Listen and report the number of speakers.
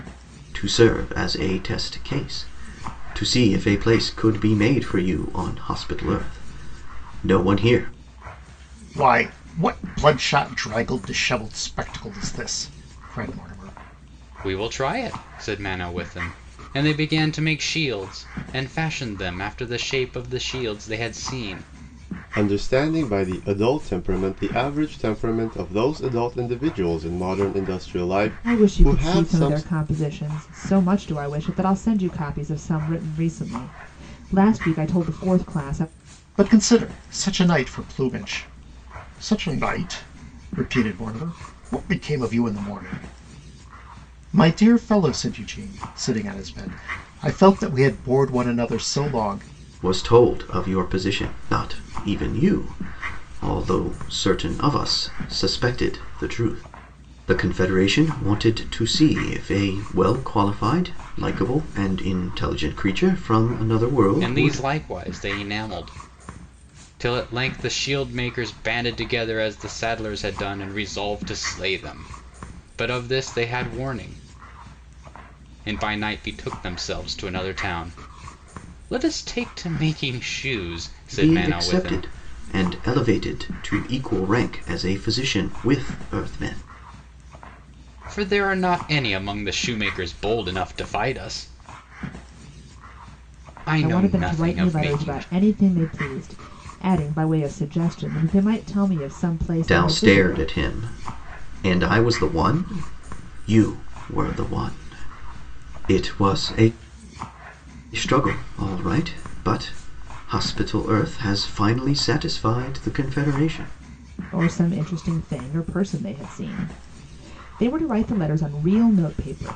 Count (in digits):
5